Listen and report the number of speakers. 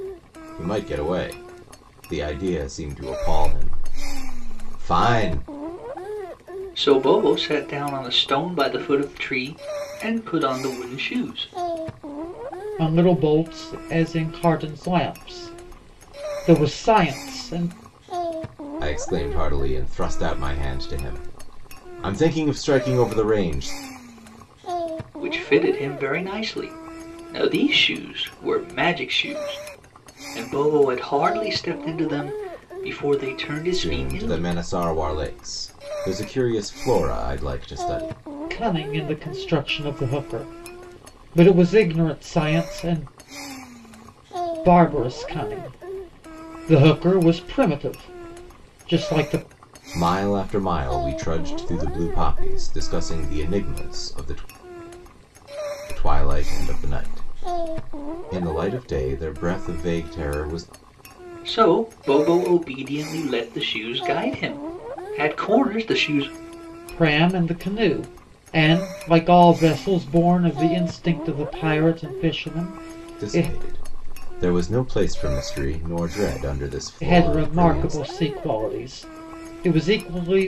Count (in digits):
3